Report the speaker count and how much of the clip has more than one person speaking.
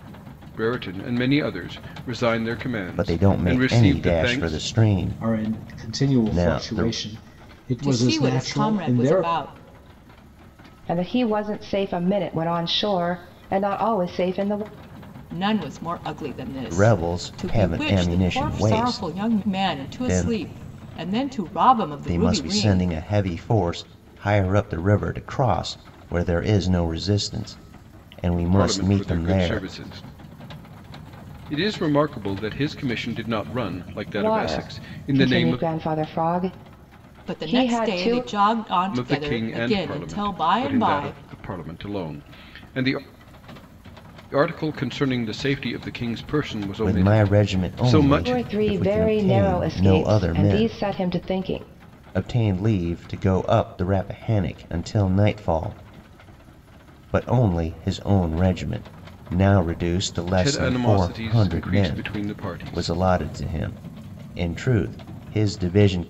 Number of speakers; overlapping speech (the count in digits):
5, about 33%